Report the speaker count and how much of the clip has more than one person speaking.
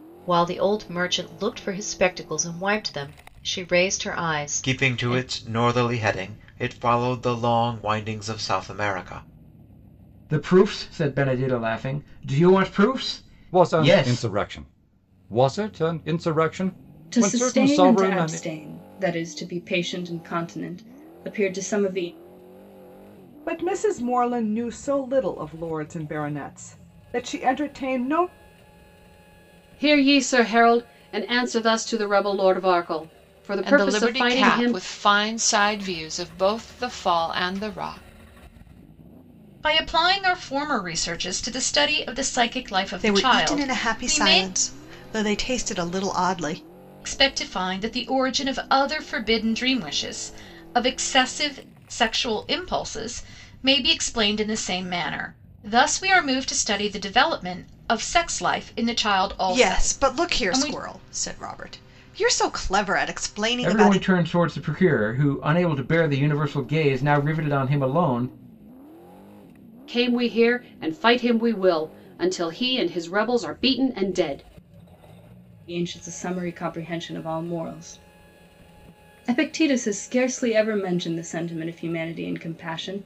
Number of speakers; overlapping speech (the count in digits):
10, about 9%